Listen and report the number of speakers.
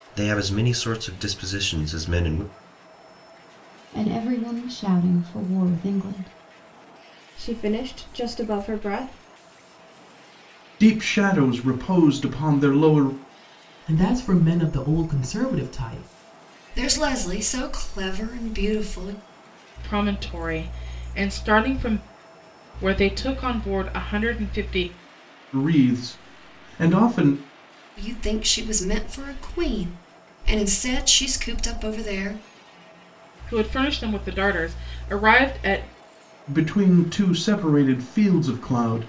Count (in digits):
7